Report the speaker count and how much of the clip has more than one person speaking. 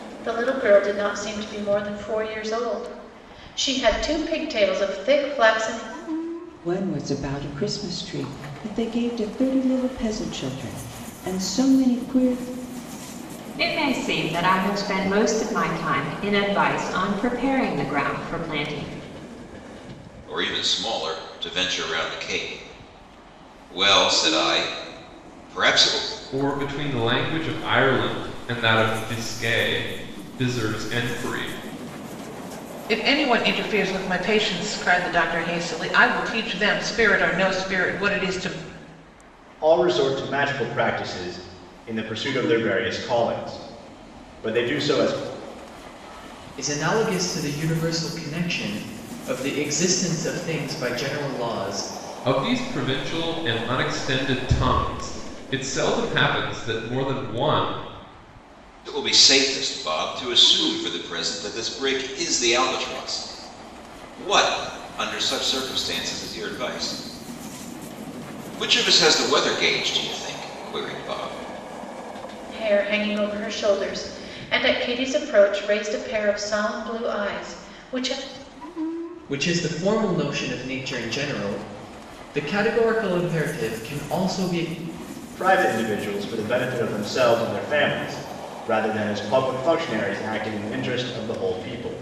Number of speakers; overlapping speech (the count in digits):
8, no overlap